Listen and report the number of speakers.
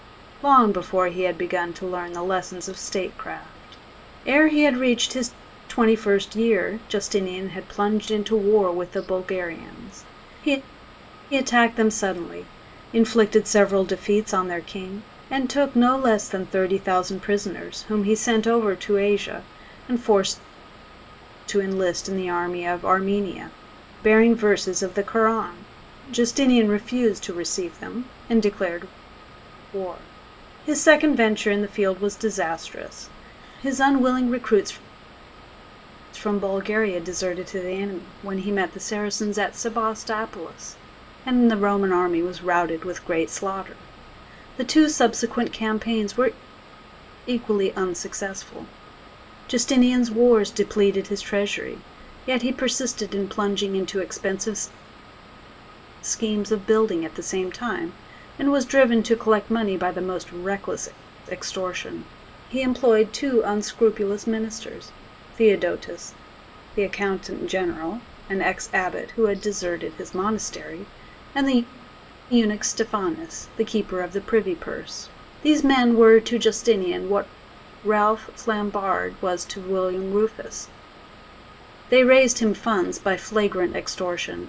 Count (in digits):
1